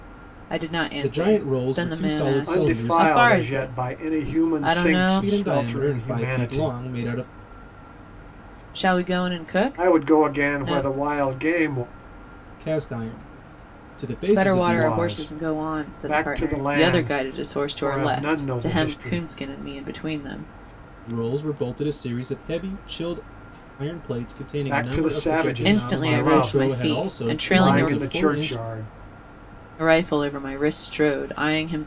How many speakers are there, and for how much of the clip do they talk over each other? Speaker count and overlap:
three, about 48%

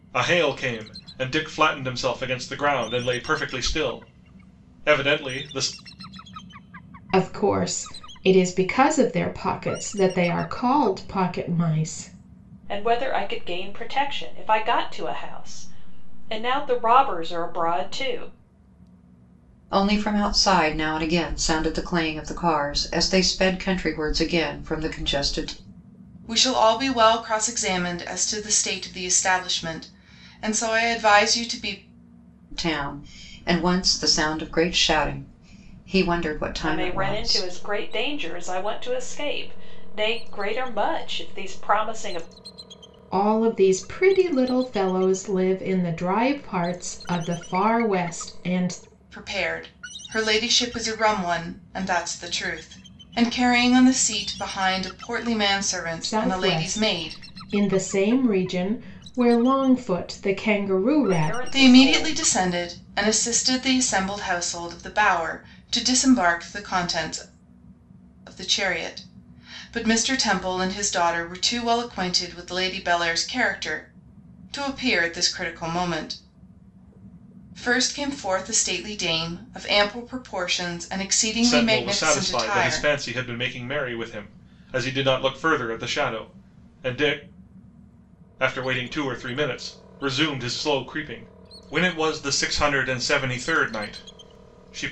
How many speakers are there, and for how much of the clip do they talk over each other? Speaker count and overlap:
five, about 5%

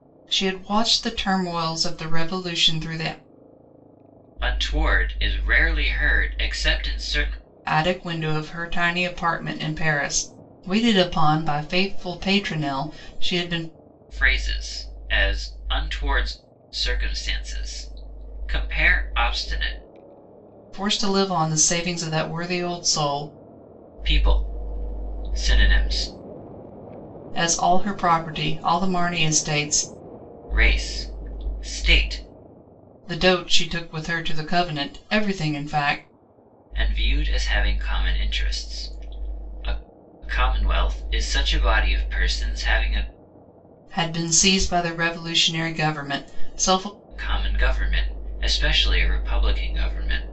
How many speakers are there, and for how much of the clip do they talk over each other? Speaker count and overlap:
two, no overlap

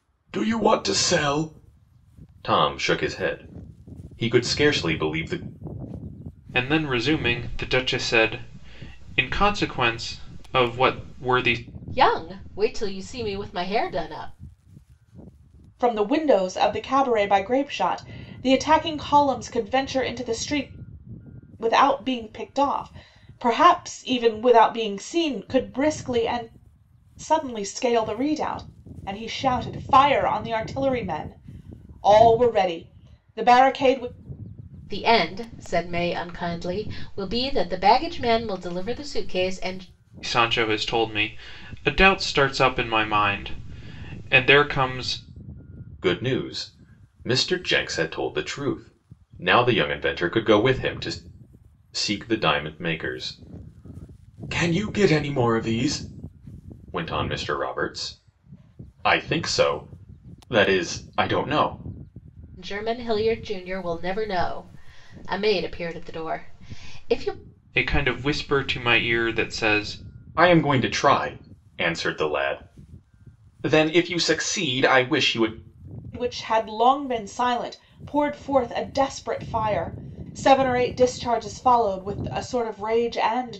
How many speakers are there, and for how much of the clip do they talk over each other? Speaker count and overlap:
four, no overlap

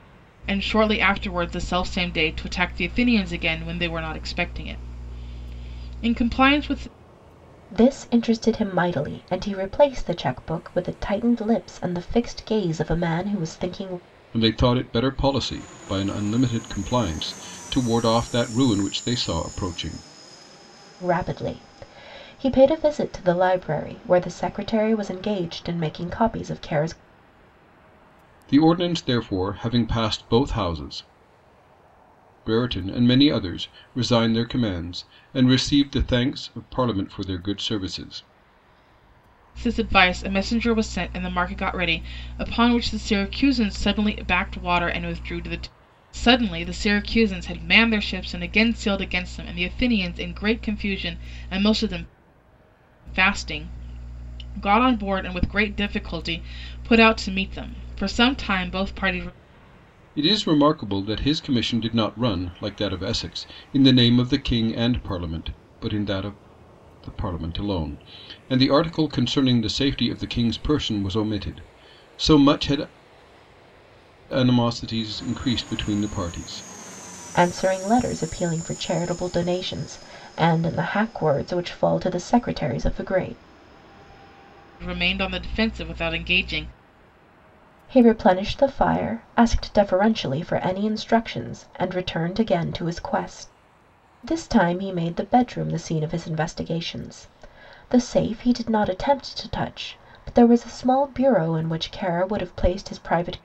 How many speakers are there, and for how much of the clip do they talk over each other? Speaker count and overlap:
three, no overlap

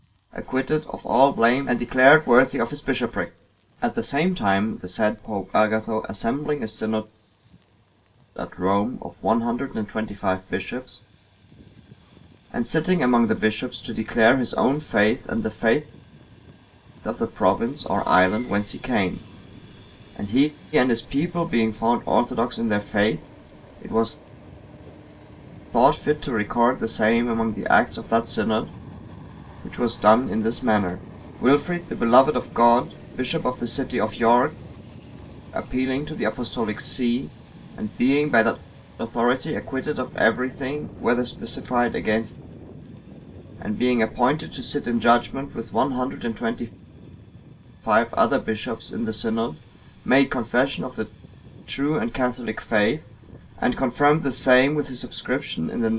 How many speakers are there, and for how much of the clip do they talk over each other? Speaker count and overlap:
one, no overlap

